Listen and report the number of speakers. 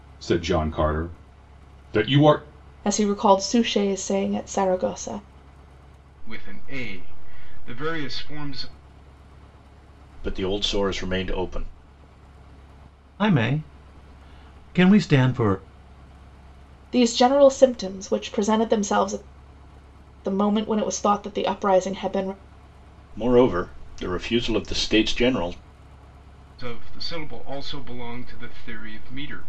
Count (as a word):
five